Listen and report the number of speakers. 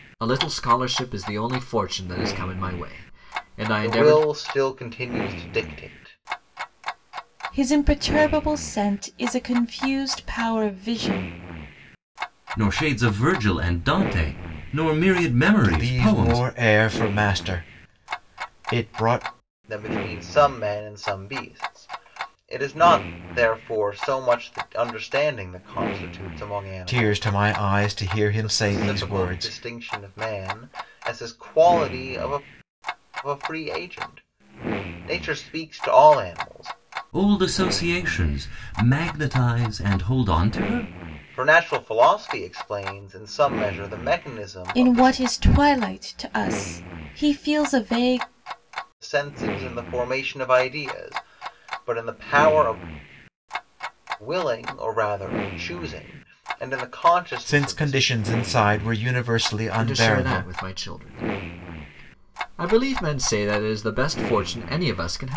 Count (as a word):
five